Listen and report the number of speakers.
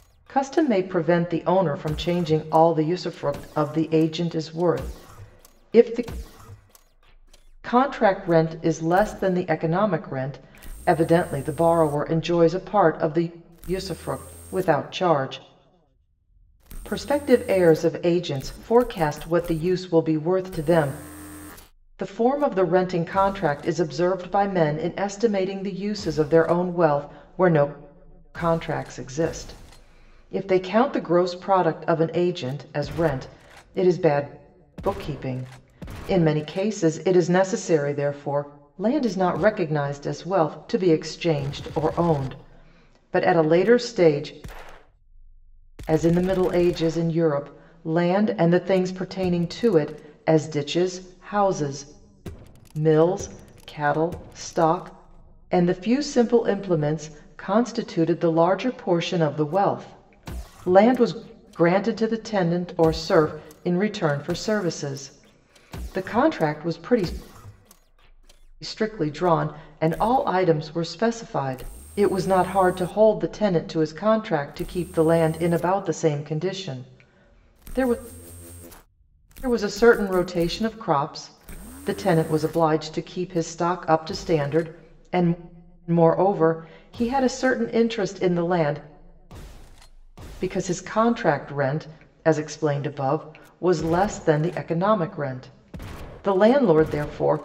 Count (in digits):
1